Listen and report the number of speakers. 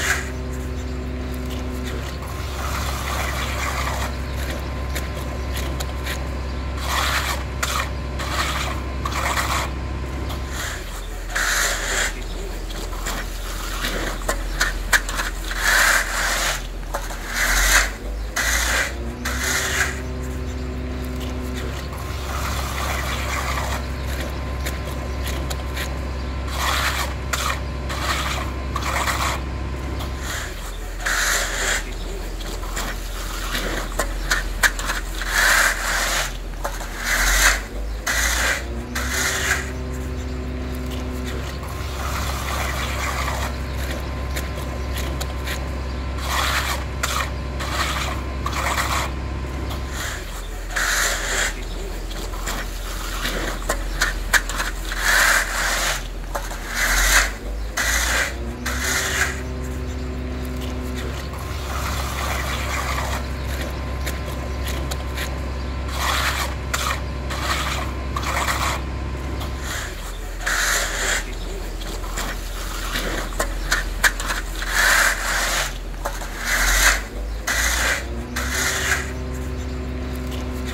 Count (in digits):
0